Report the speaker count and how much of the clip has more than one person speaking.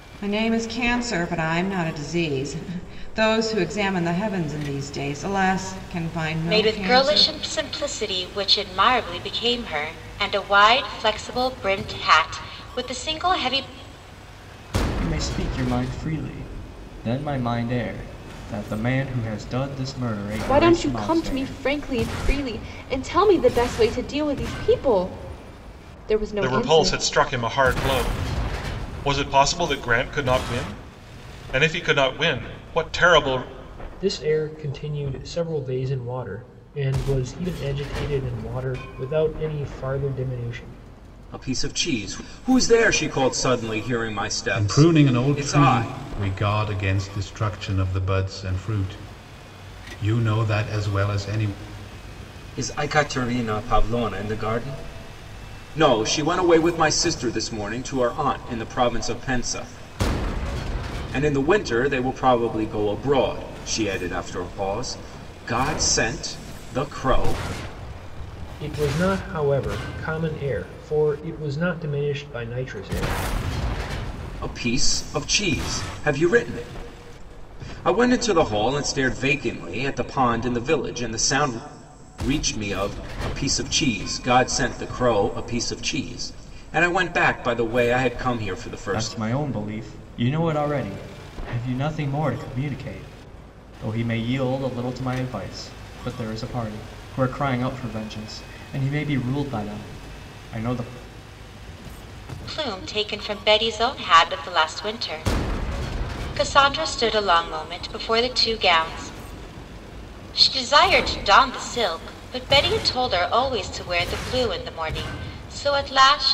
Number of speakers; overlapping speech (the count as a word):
eight, about 4%